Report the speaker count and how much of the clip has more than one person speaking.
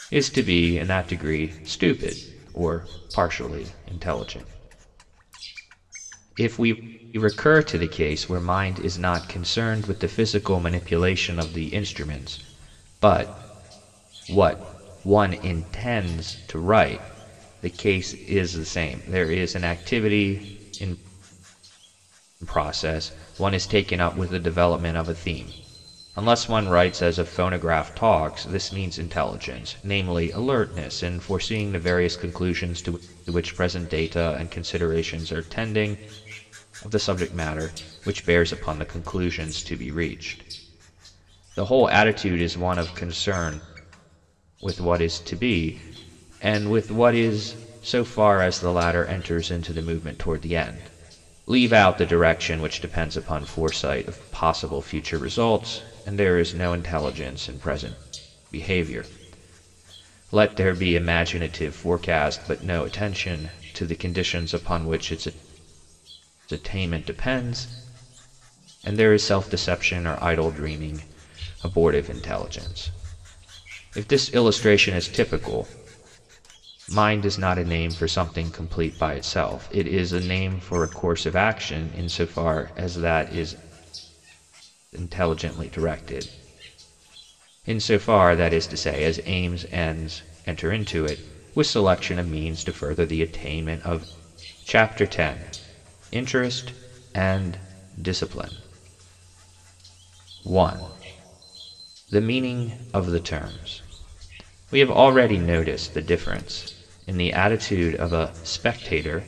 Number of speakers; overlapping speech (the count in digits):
1, no overlap